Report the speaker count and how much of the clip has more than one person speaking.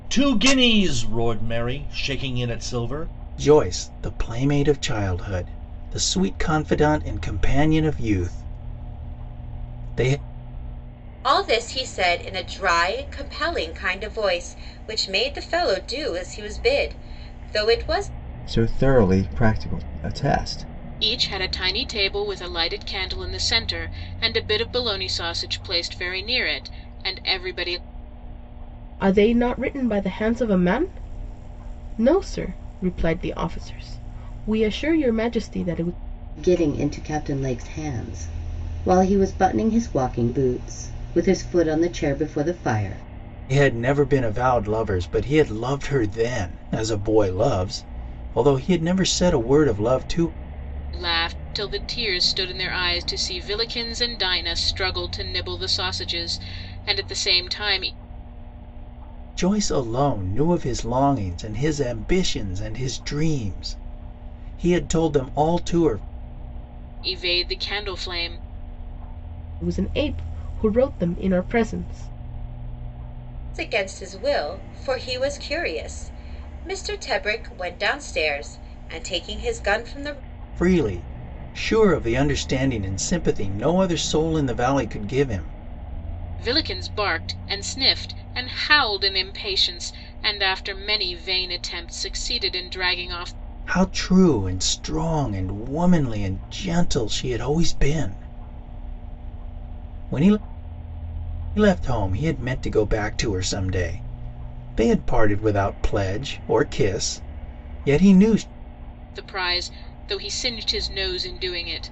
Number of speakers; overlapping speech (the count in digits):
7, no overlap